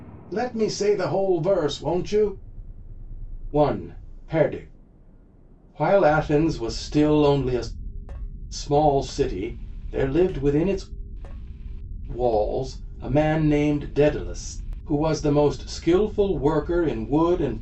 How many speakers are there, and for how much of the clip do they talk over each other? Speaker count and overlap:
1, no overlap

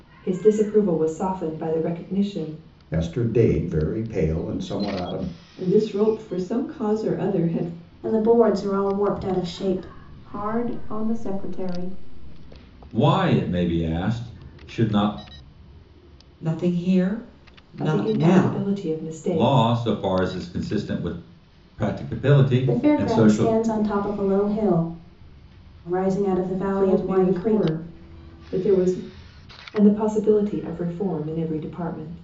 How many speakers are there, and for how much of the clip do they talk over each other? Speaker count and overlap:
7, about 10%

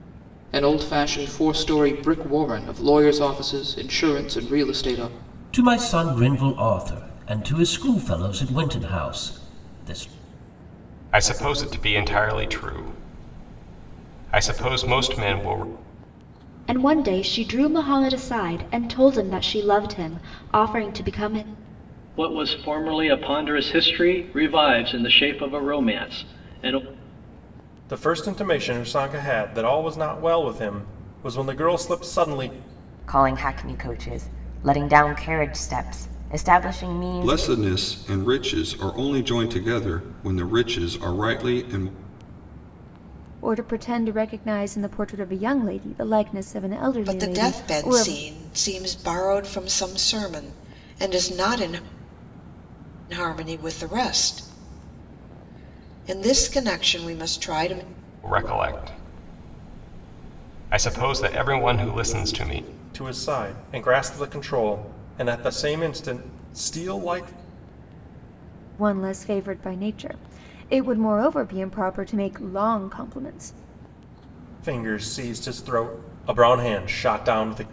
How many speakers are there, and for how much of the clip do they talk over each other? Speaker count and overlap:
10, about 2%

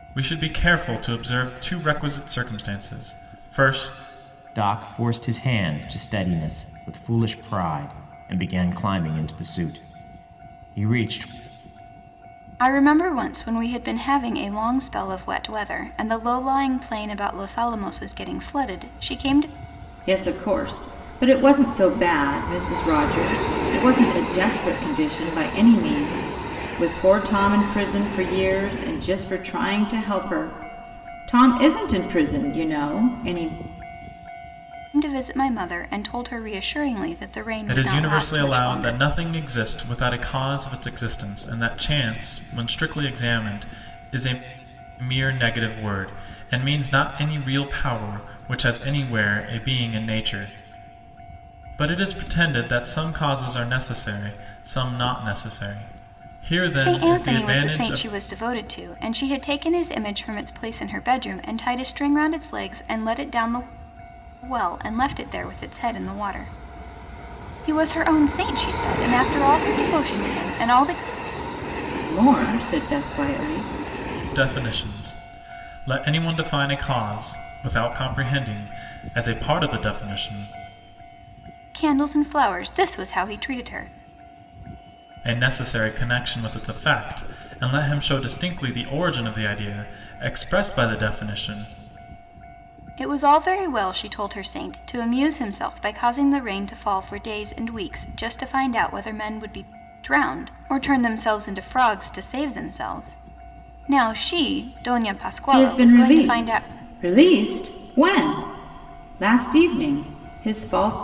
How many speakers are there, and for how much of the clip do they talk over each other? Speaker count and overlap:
4, about 4%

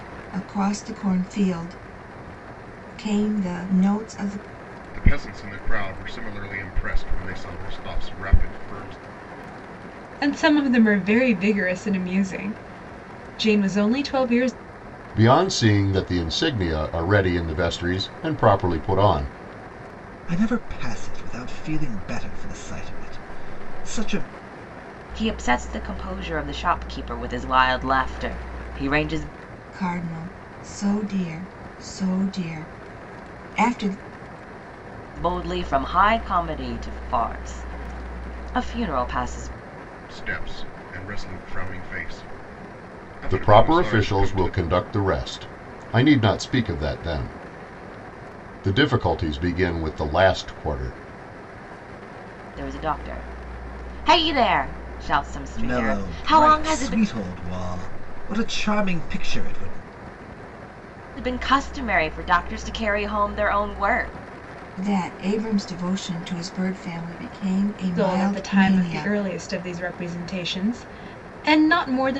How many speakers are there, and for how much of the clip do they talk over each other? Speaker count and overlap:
6, about 5%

